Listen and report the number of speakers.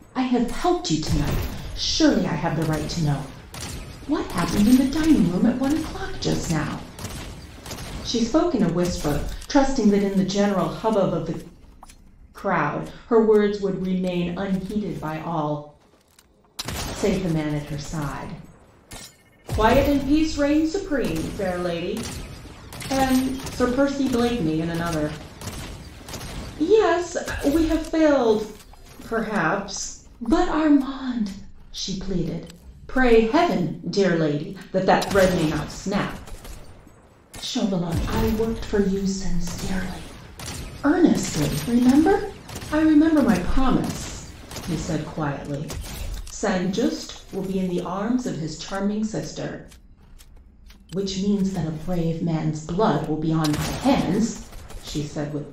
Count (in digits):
1